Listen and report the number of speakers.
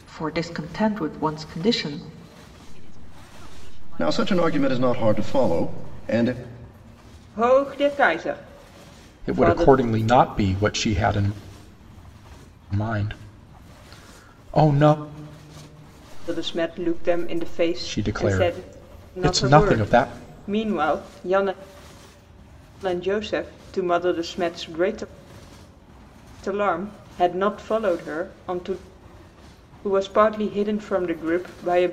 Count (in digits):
5